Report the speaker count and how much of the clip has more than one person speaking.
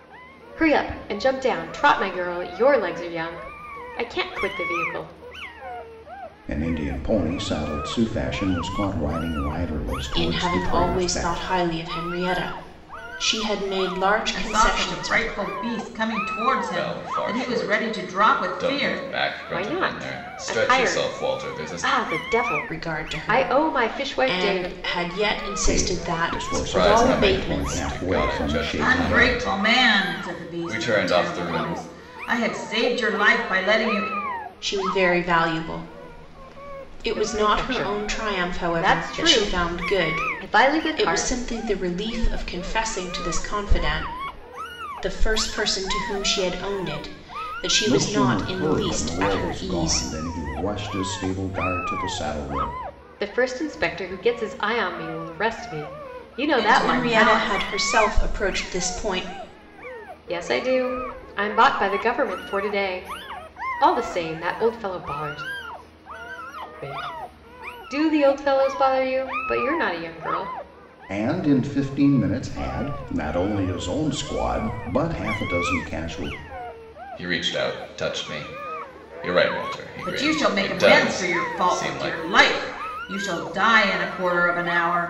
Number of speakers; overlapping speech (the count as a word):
five, about 30%